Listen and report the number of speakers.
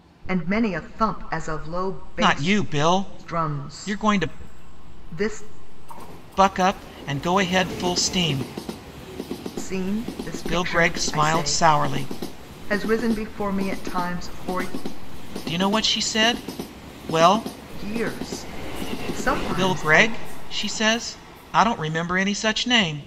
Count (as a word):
two